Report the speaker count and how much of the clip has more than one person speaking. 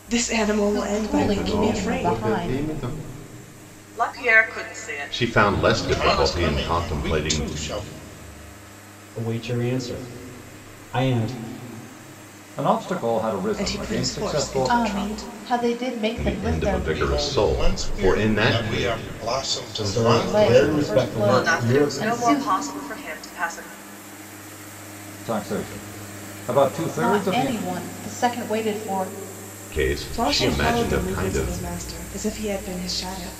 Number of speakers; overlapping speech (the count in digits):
8, about 44%